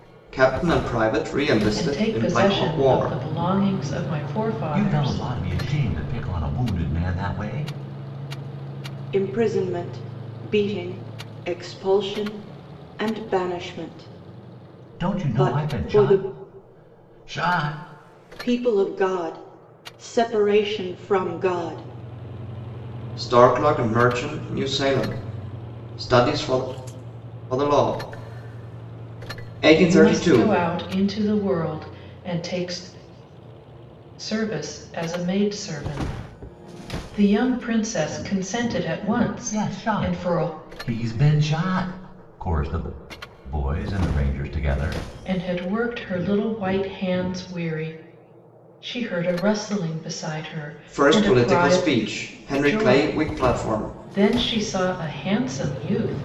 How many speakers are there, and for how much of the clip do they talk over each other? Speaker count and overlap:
four, about 13%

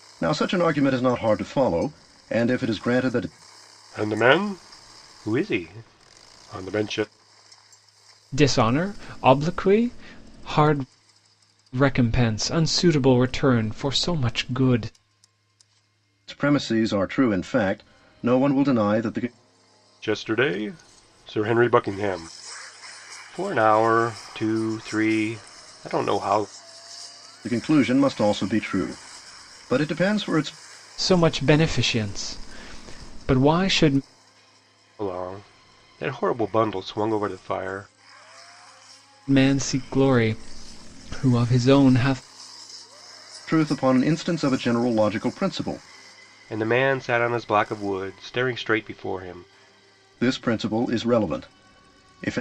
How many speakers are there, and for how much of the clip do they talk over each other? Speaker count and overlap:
three, no overlap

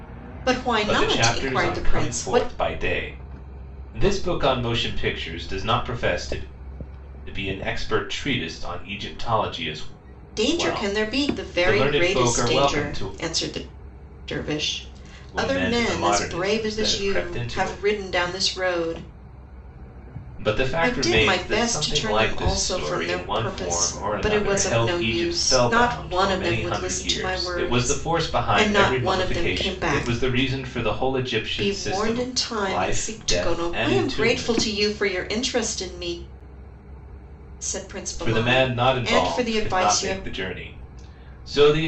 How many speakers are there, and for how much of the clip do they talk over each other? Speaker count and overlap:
two, about 49%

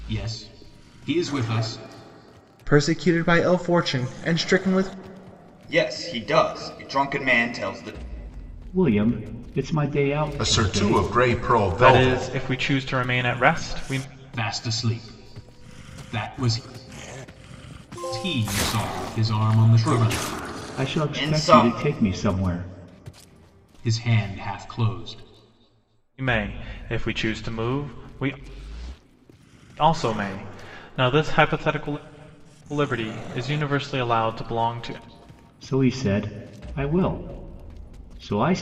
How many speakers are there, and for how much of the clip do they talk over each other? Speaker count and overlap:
six, about 8%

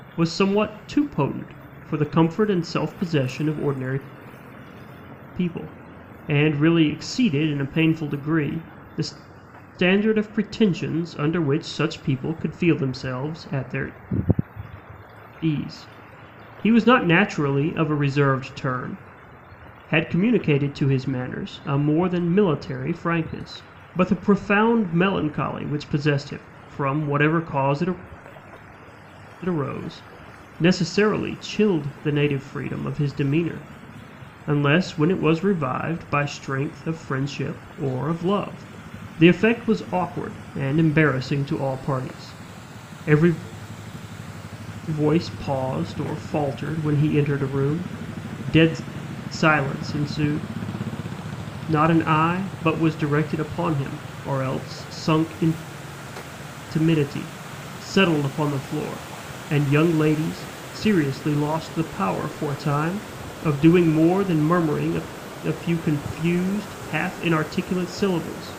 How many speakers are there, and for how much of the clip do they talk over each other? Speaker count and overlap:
one, no overlap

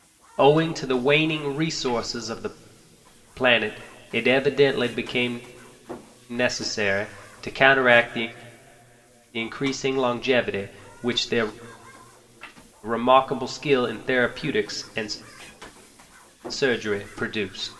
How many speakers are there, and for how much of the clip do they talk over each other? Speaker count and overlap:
one, no overlap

